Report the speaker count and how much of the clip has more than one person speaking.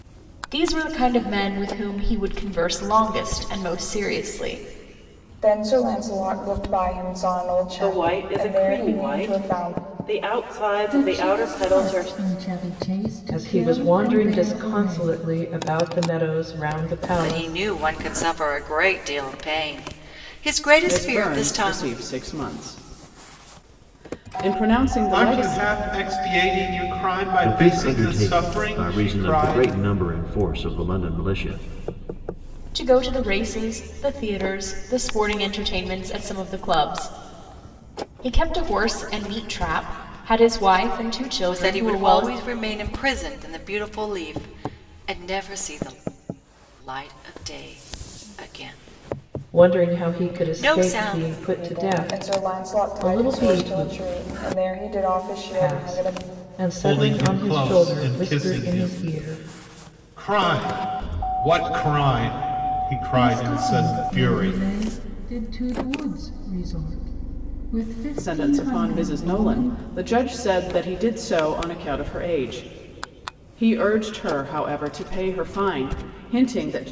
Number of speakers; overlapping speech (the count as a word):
nine, about 28%